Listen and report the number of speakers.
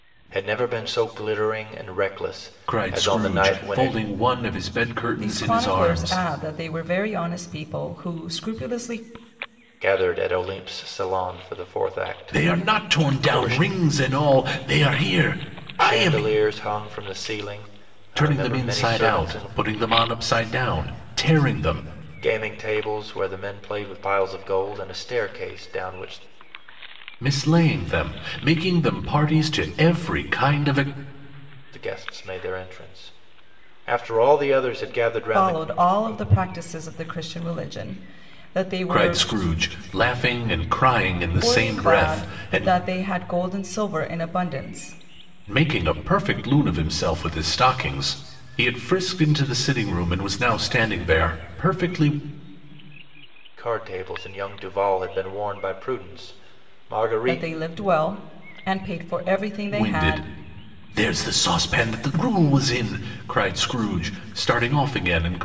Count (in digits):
3